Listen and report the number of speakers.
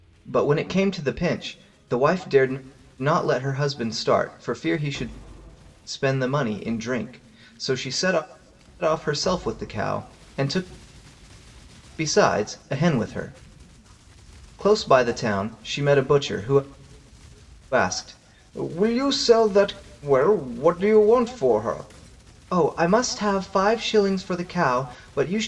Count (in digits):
1